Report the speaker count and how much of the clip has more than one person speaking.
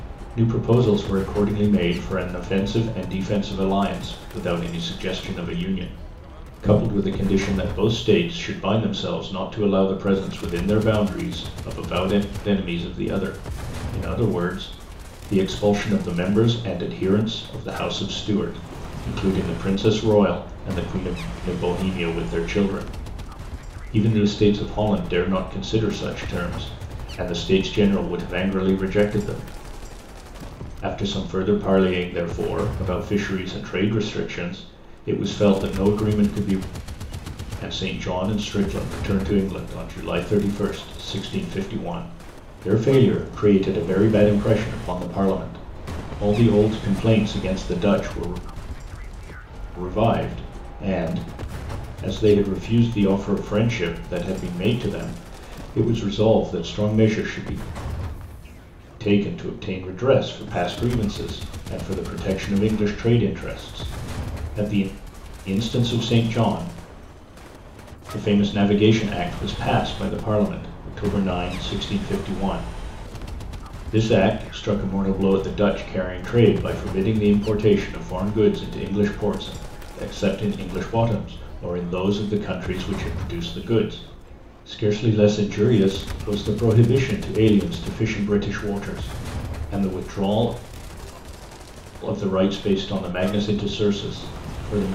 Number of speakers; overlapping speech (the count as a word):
one, no overlap